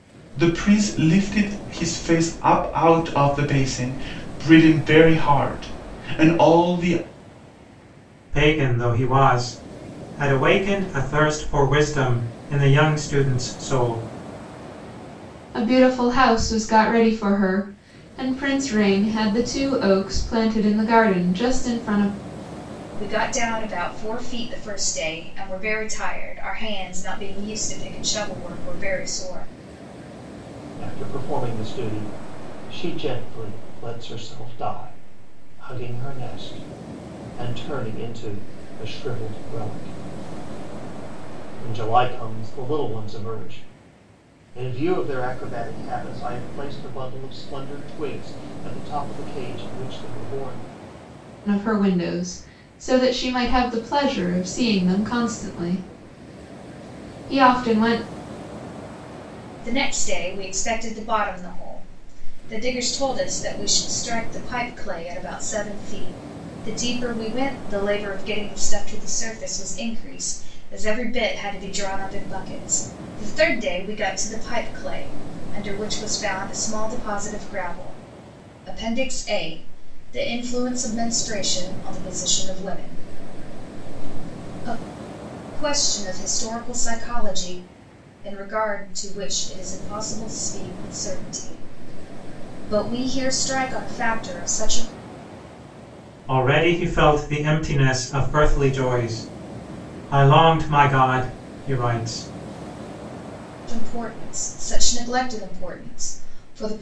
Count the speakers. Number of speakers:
5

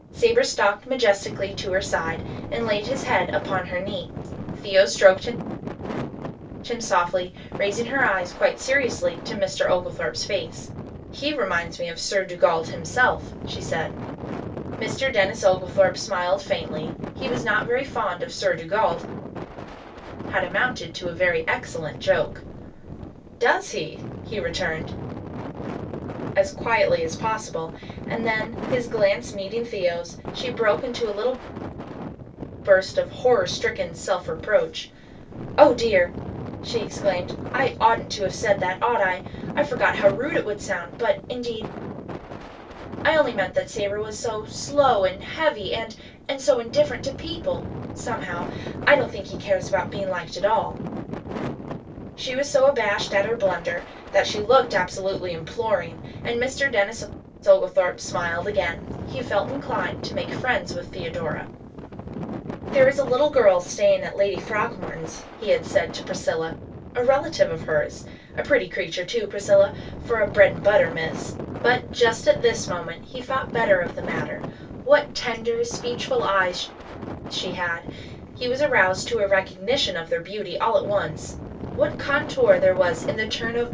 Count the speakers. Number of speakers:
1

